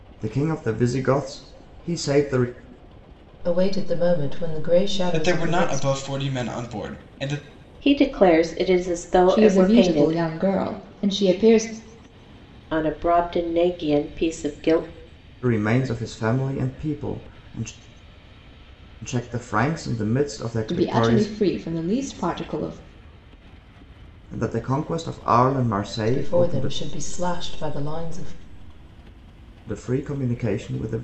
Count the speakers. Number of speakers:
5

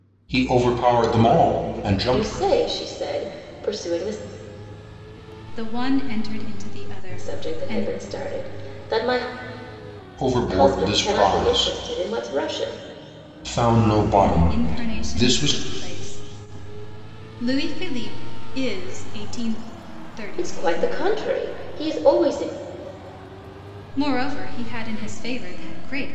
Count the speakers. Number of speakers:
3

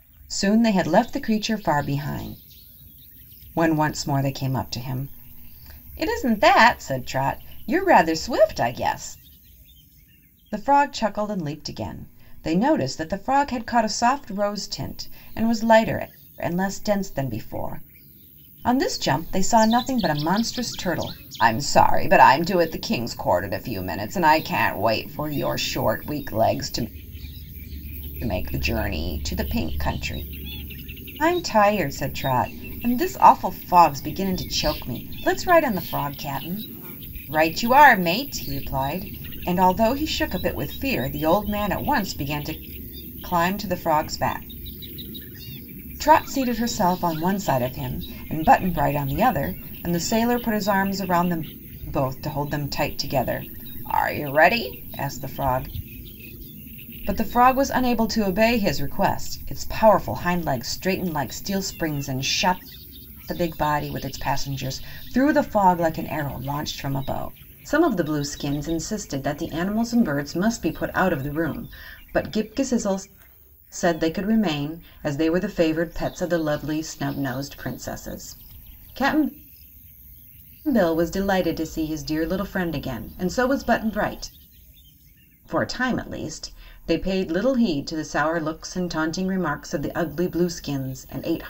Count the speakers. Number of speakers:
1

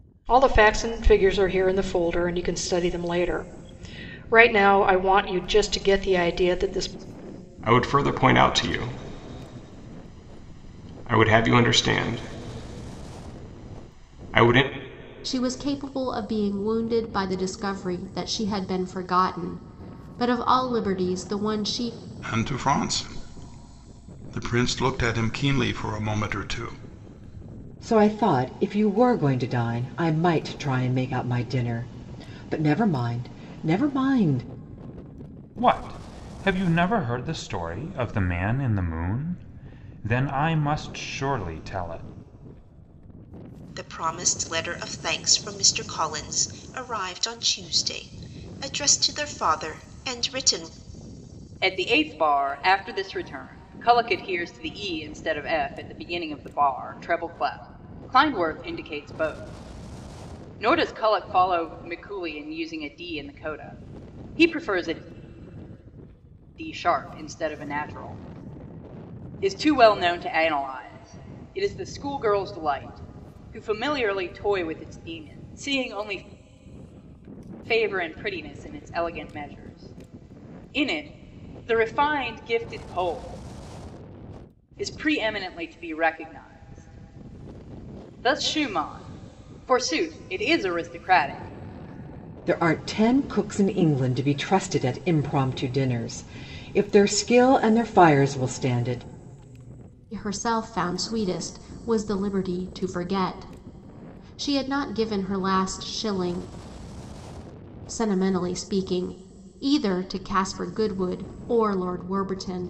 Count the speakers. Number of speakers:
8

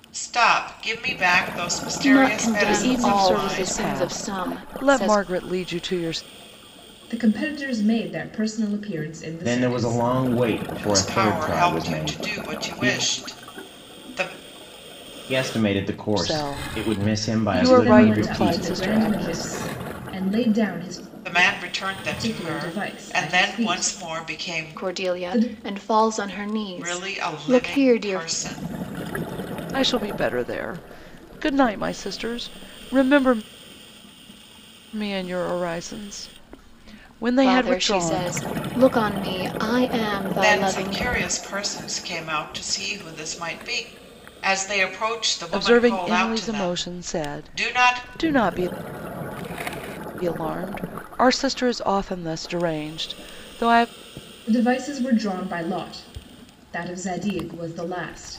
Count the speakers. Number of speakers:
5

